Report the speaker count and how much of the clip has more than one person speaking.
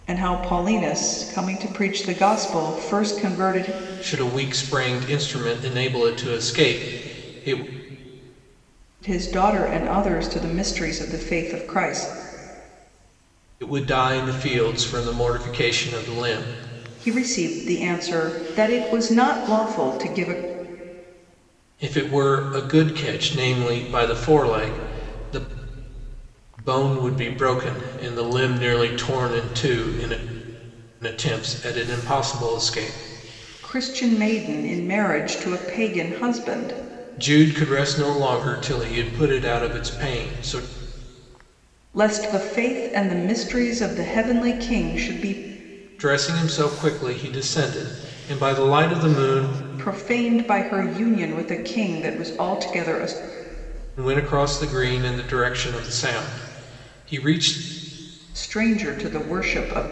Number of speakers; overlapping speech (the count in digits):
2, no overlap